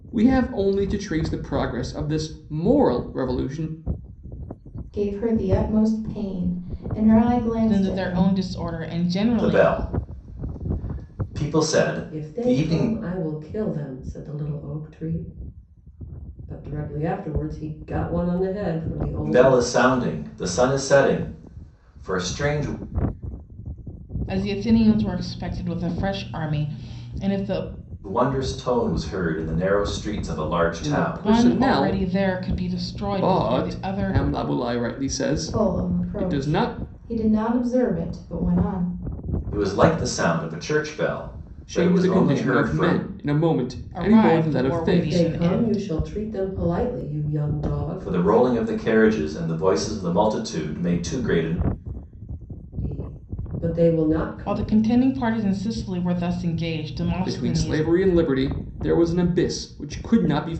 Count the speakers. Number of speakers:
5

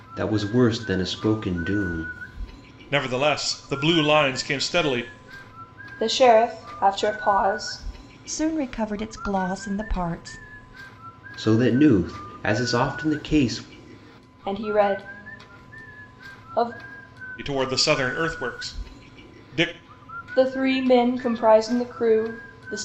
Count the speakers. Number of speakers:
4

